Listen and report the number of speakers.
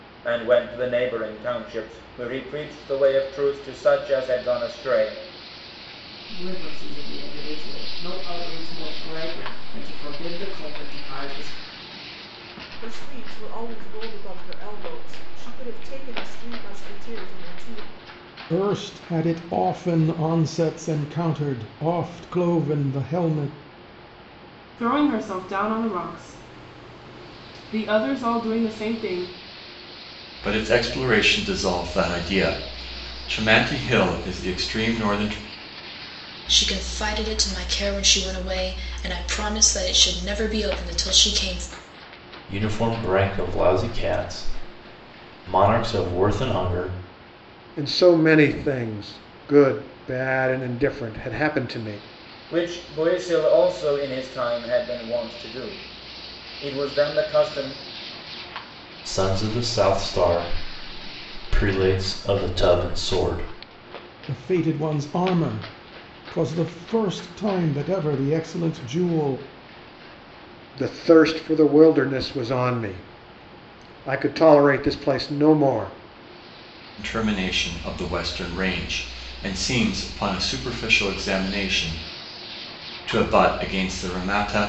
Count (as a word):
nine